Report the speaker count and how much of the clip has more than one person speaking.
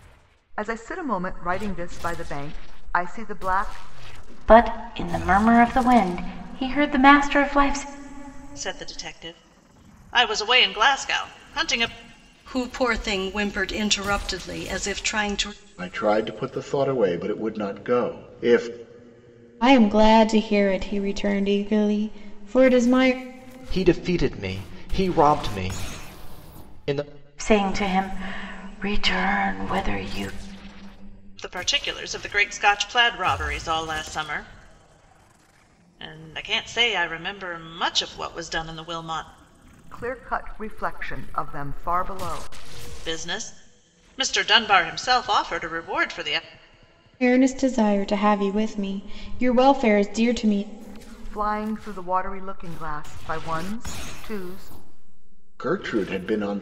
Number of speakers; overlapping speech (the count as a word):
seven, no overlap